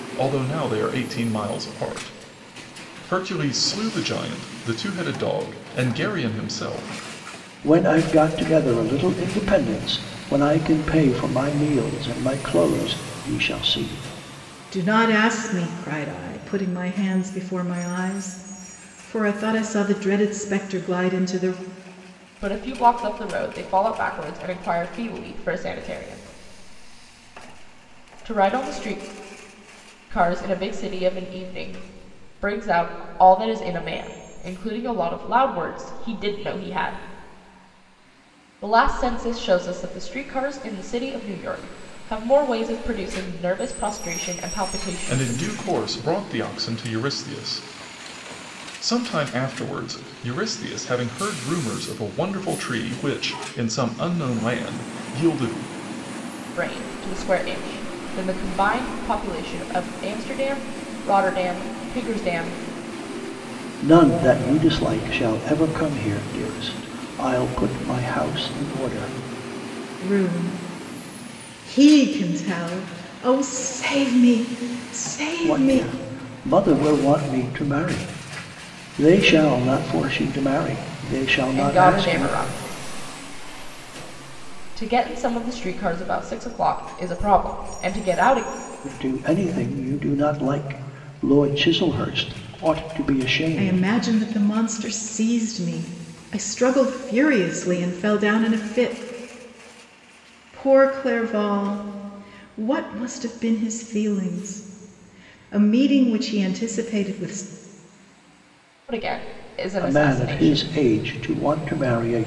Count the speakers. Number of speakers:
4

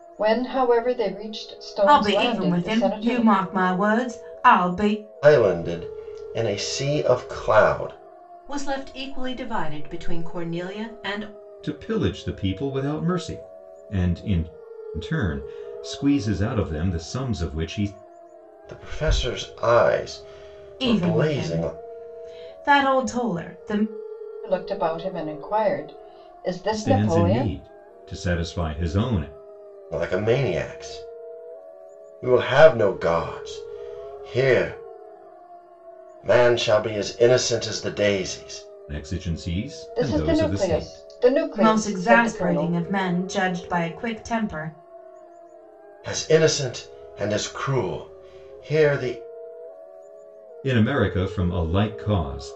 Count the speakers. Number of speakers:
5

